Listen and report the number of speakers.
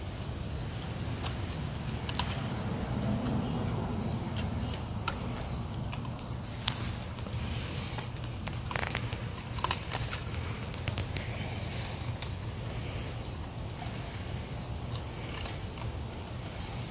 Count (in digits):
0